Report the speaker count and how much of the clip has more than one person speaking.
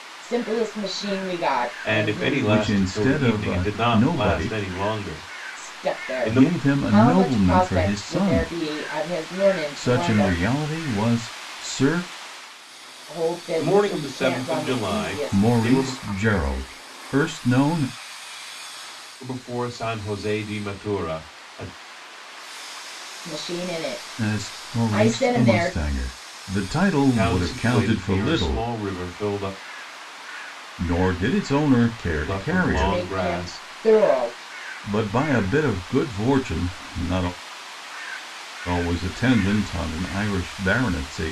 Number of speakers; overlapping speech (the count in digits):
3, about 31%